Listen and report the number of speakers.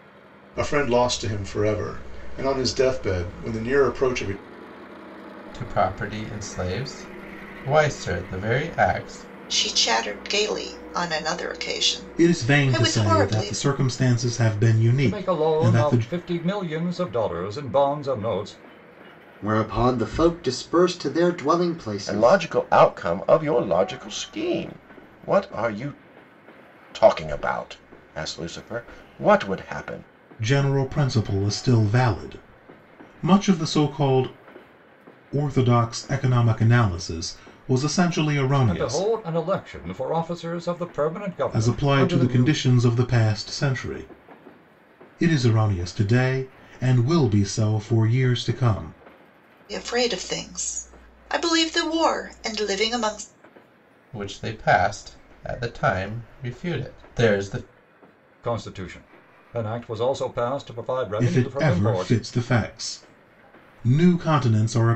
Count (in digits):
7